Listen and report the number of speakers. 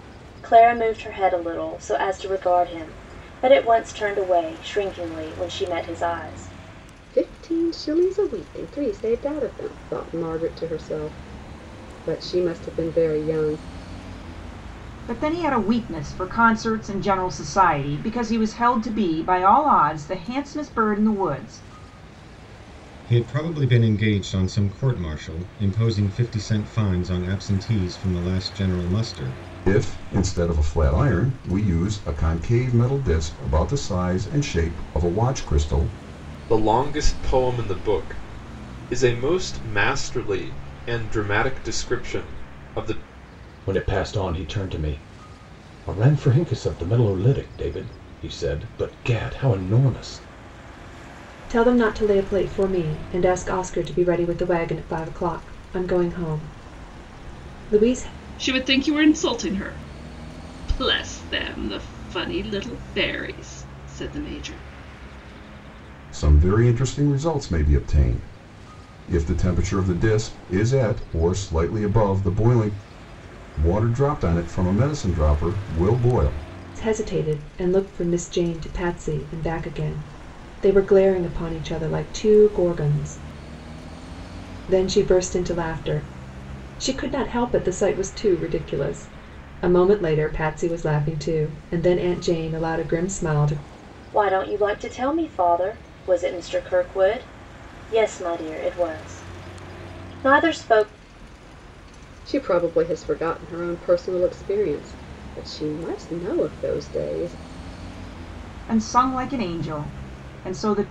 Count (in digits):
9